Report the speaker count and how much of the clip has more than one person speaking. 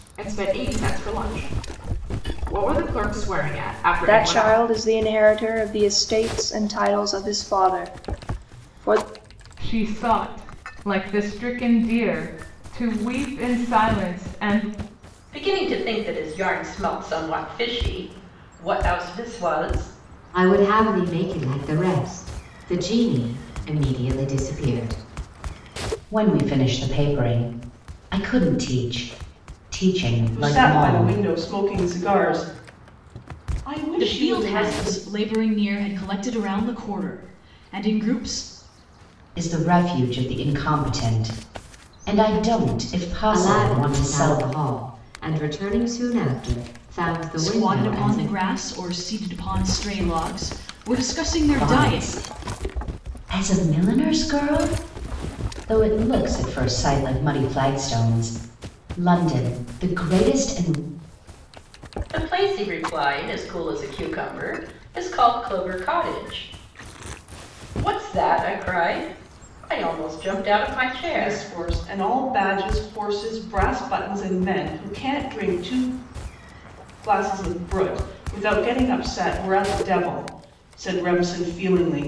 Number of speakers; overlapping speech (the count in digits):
8, about 7%